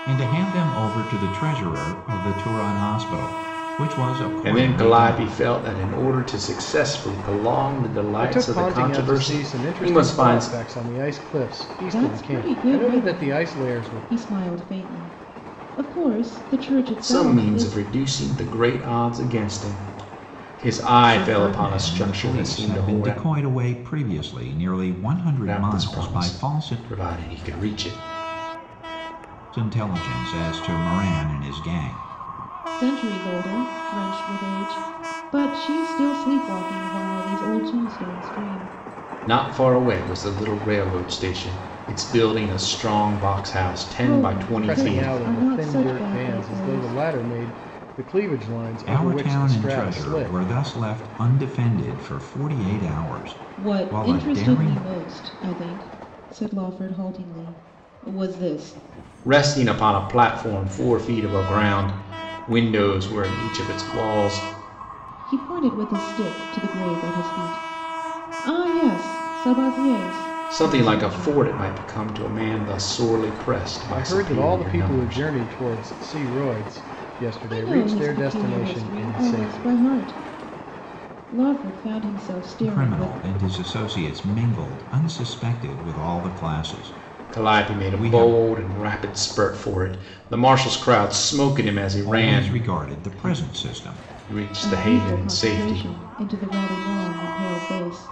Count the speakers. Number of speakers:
4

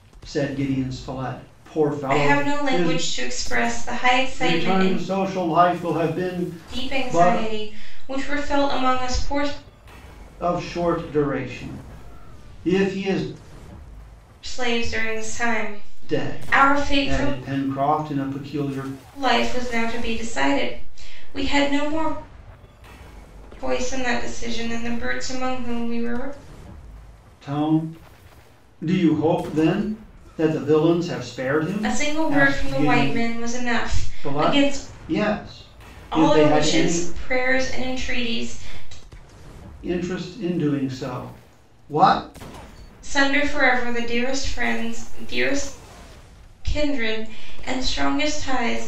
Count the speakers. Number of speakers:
2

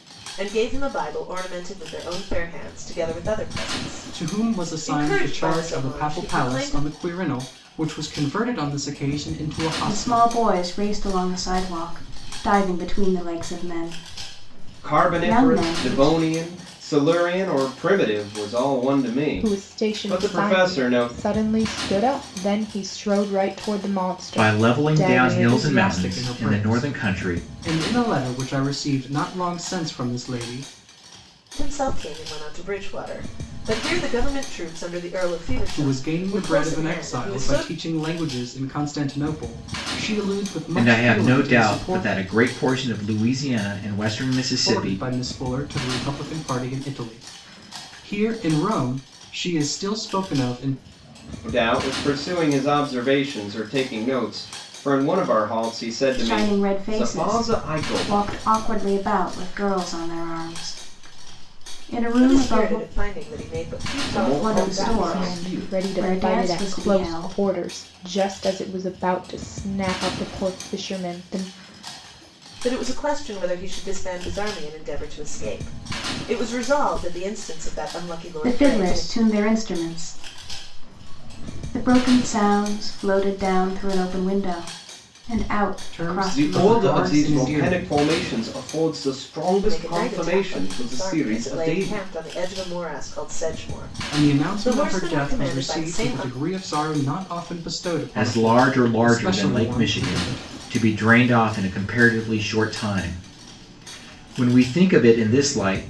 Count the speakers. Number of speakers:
6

